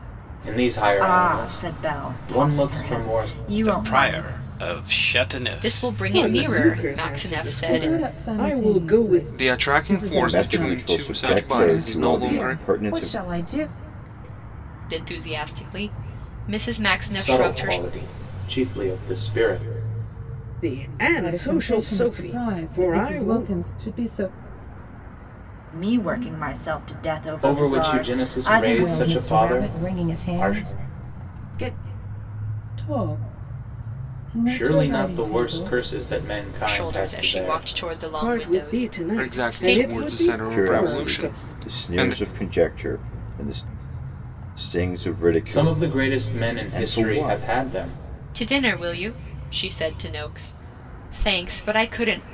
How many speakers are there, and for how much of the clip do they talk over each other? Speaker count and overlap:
nine, about 49%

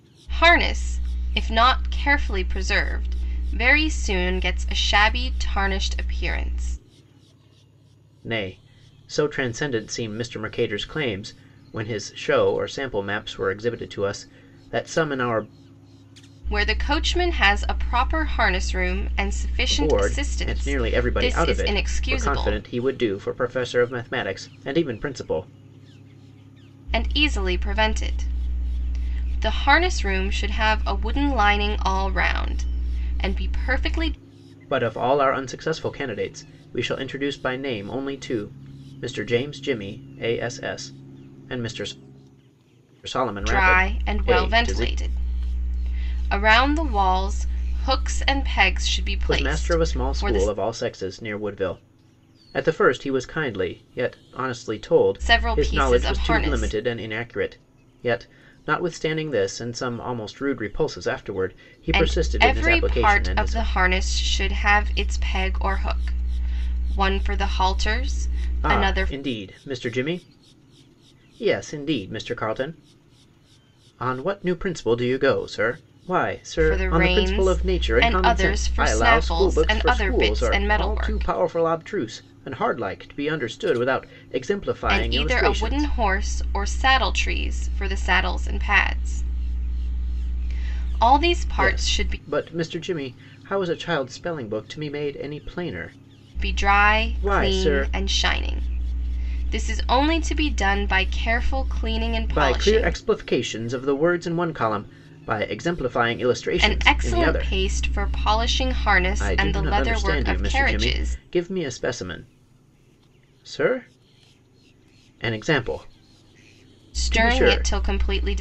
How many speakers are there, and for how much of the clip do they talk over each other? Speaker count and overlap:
two, about 20%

